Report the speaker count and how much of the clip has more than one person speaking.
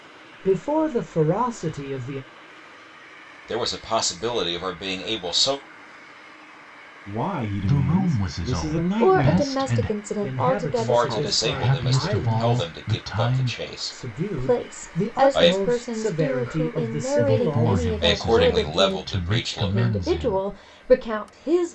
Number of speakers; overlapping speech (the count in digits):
5, about 56%